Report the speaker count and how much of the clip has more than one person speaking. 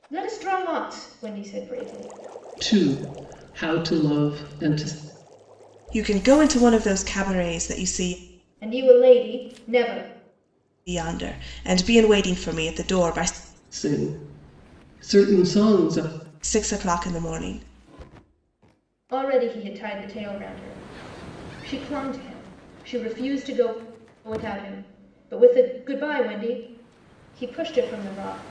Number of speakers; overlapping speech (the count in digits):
3, no overlap